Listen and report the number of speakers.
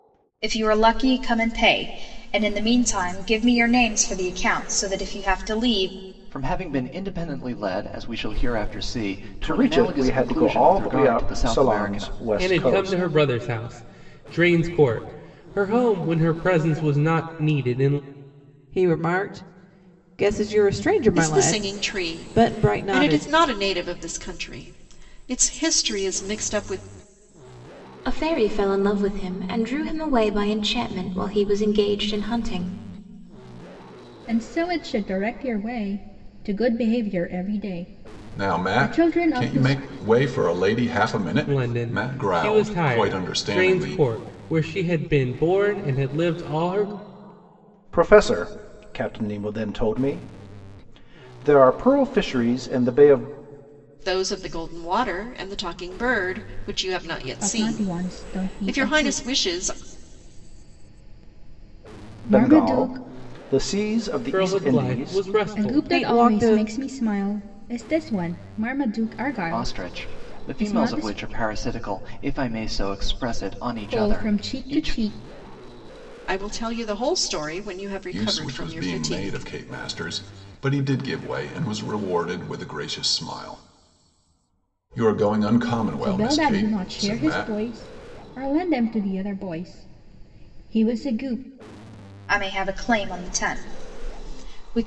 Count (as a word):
nine